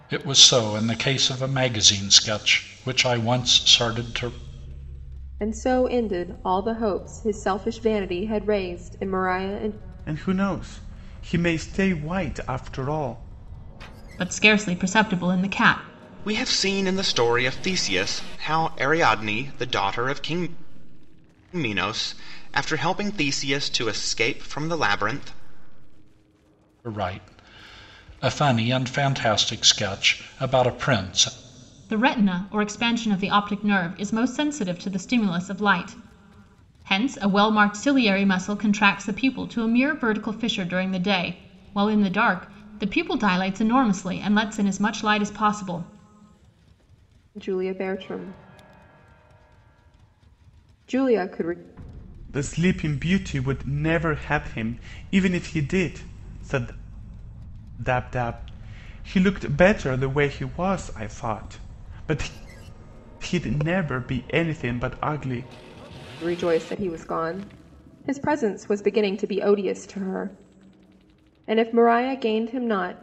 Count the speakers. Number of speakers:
five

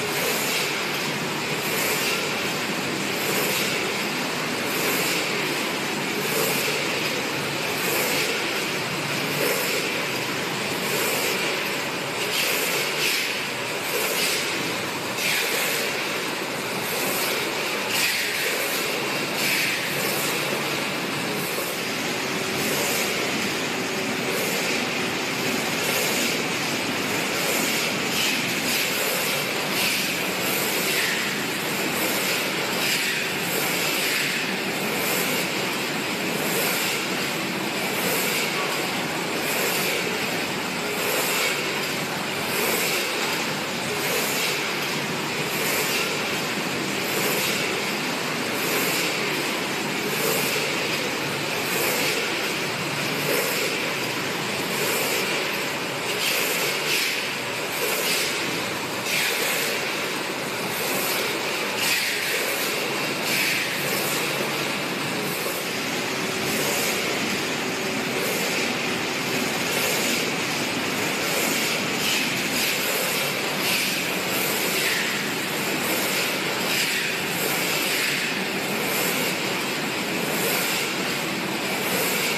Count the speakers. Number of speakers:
zero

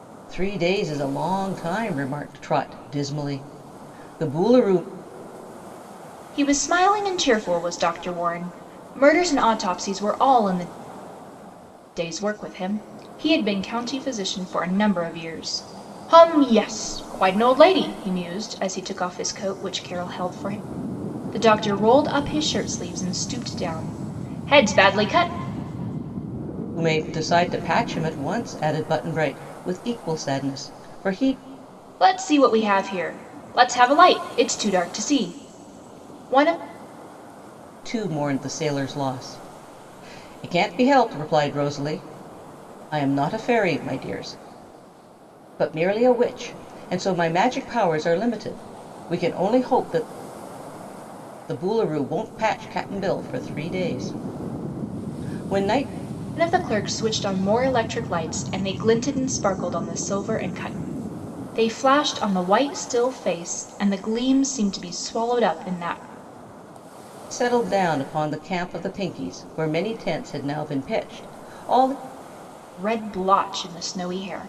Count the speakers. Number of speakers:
two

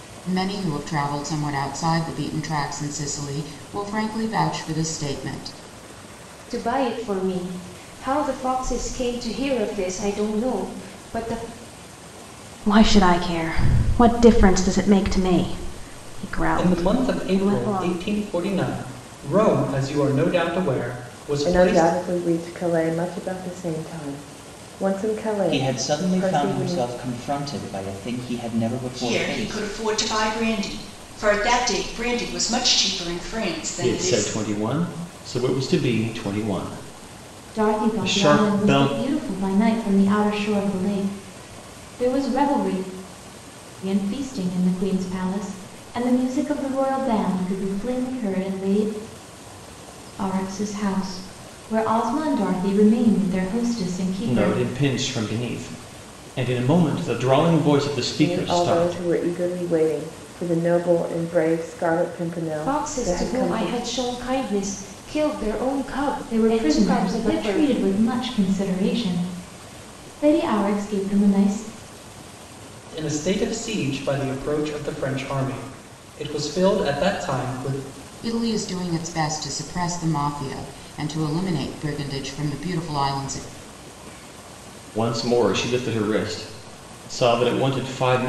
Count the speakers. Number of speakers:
nine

